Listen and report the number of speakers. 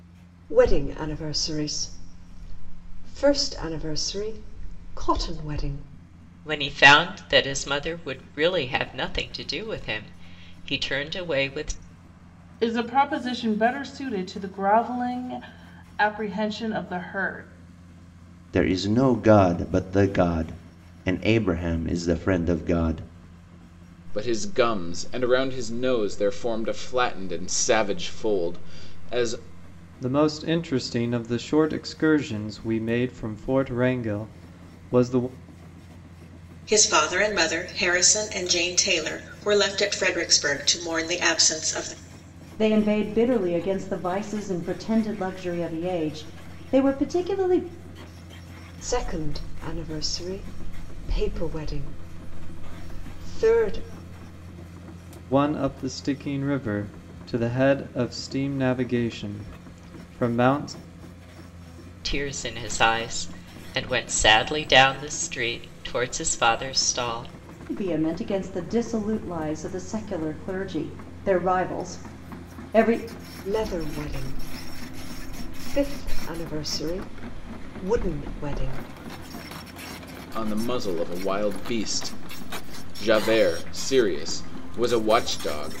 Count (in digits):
8